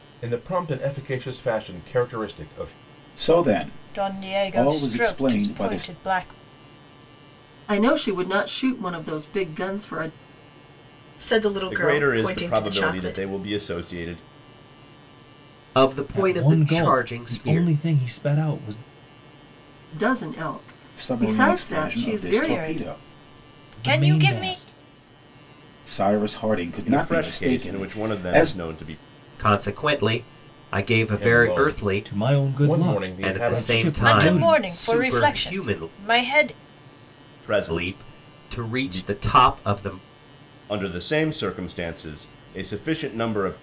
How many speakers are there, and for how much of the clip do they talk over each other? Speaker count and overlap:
eight, about 37%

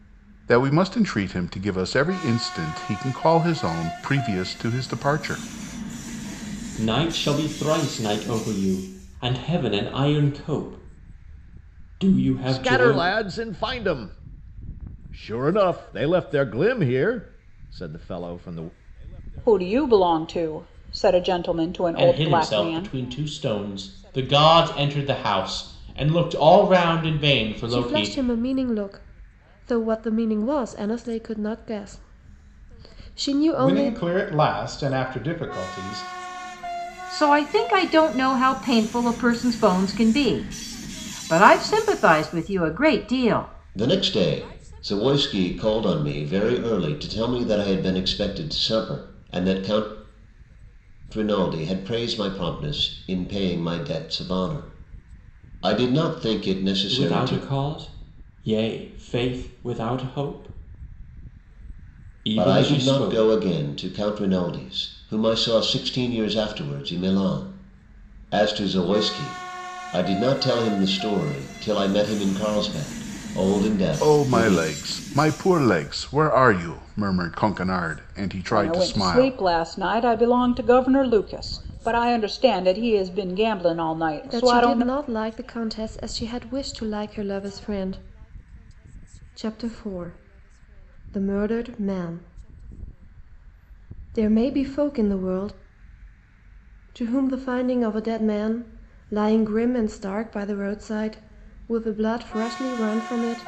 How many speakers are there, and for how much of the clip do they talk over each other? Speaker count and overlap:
nine, about 6%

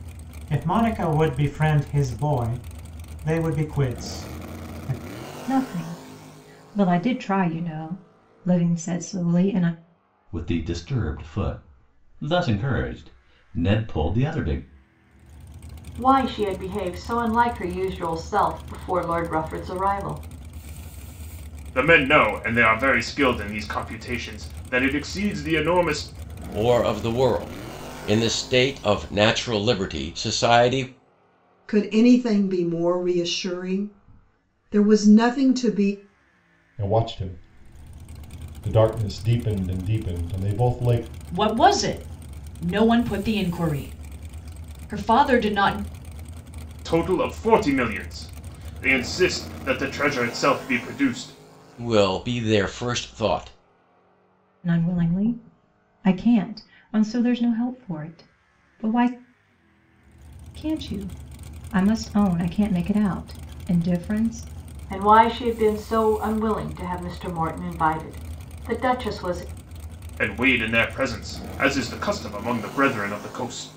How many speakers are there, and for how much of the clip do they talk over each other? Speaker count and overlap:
nine, no overlap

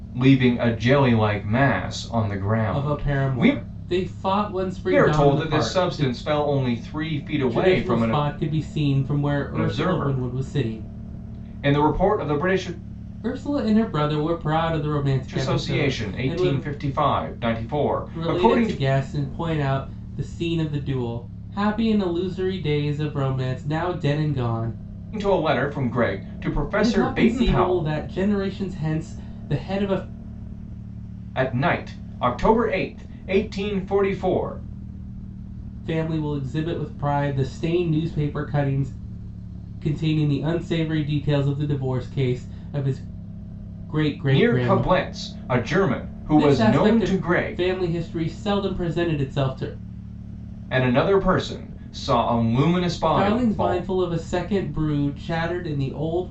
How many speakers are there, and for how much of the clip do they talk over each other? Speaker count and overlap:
two, about 19%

